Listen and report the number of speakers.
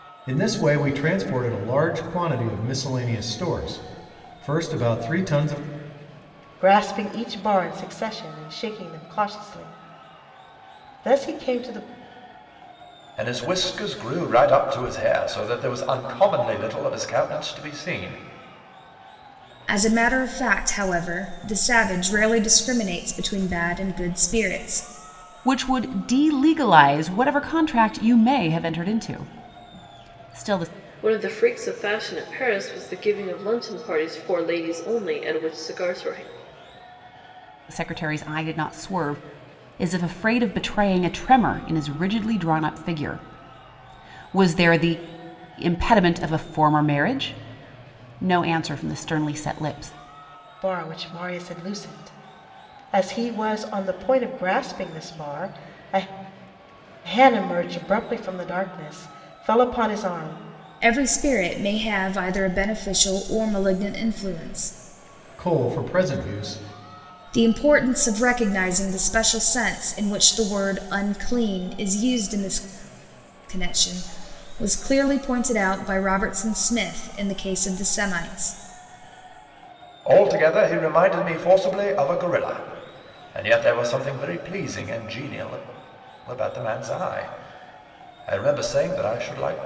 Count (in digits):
6